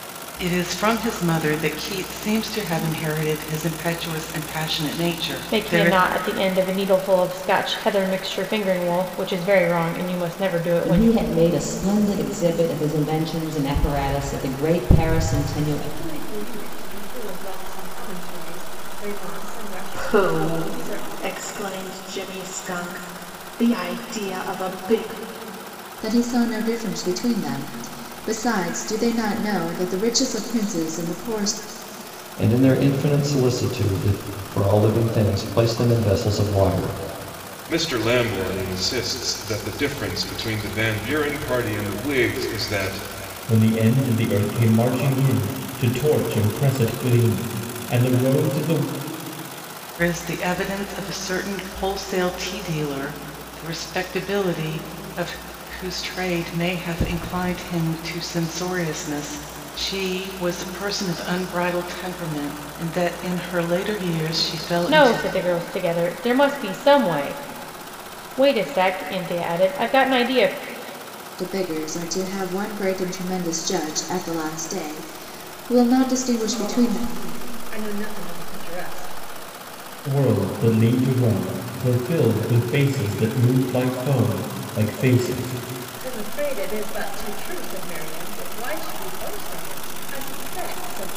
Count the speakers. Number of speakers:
9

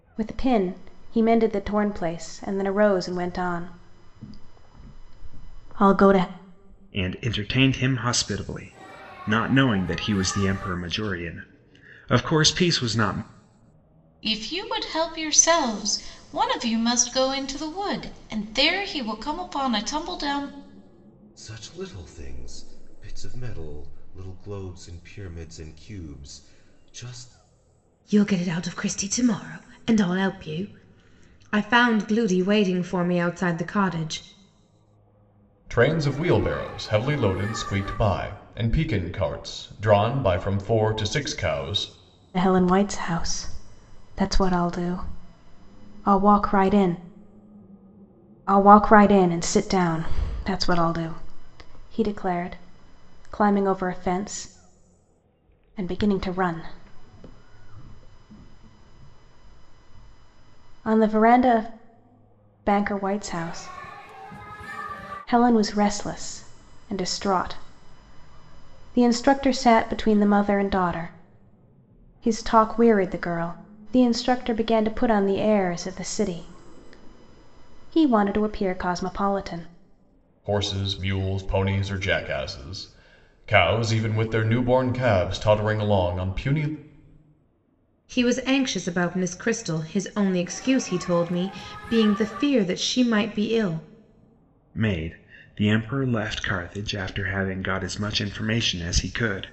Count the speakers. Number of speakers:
6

